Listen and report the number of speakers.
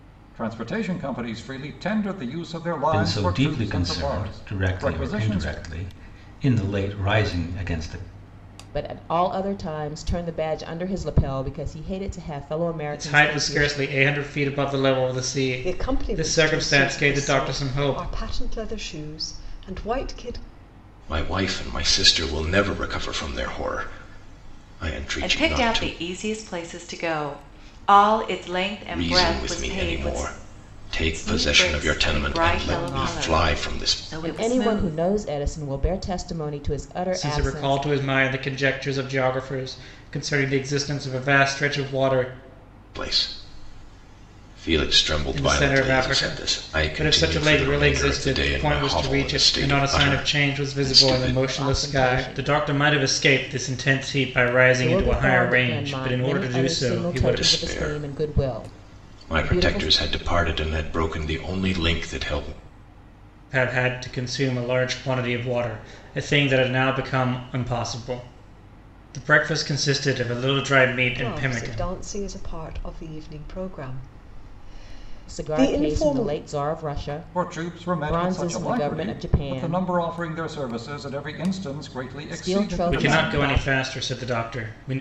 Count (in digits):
7